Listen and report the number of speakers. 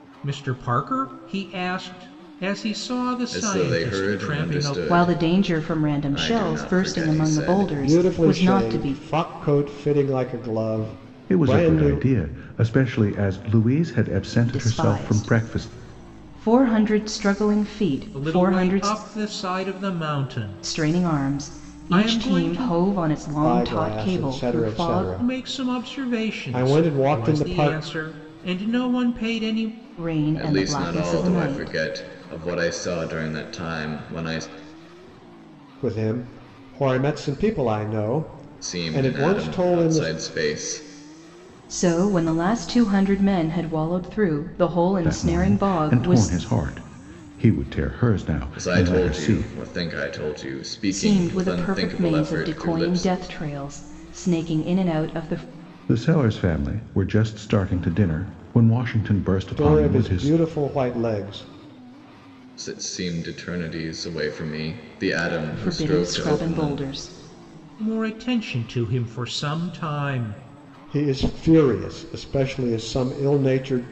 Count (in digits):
5